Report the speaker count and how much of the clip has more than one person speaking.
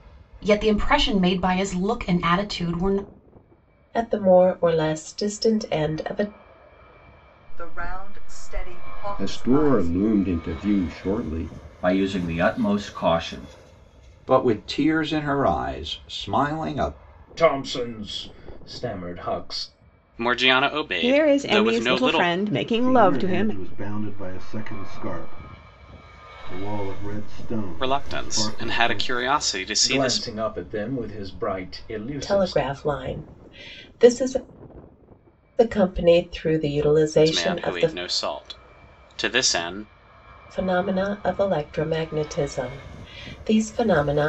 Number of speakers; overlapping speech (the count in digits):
10, about 14%